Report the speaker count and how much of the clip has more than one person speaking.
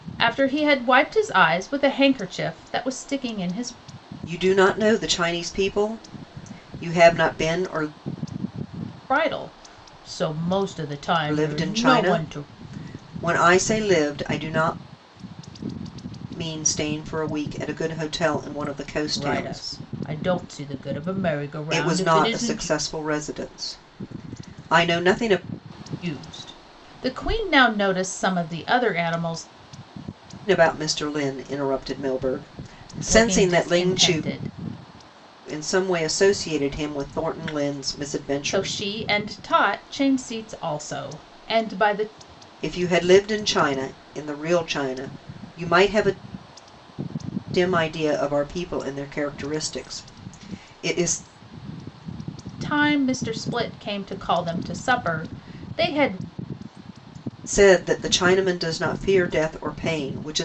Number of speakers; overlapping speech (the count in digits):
2, about 7%